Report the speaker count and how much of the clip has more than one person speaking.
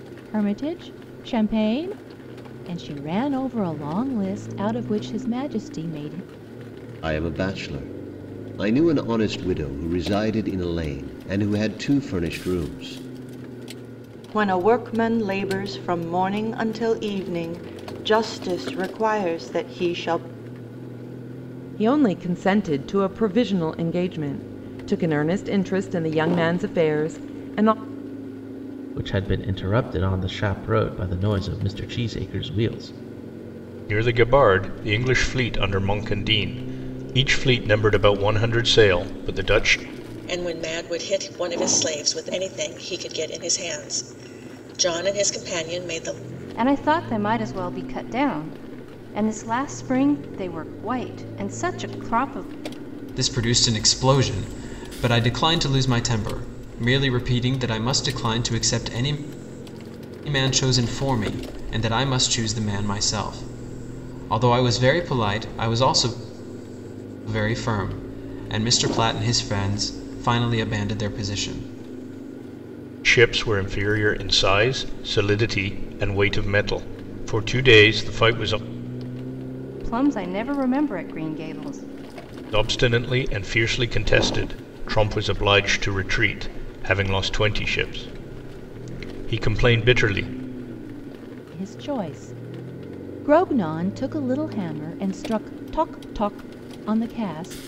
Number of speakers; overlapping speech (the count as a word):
nine, no overlap